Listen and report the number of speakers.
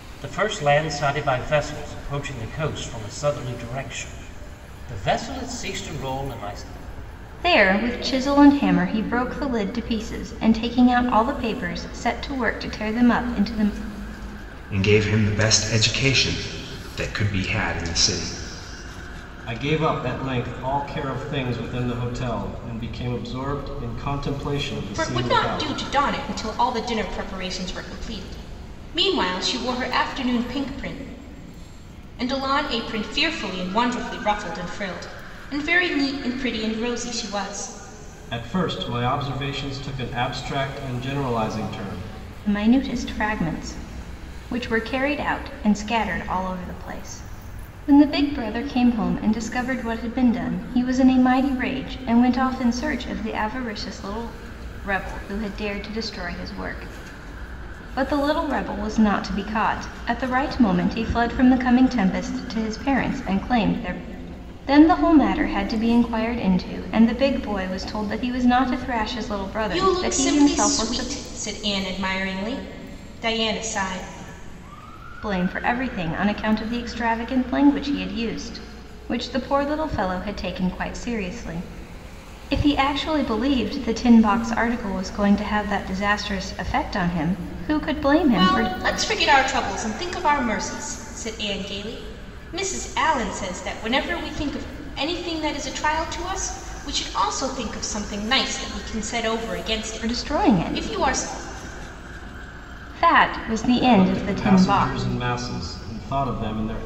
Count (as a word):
five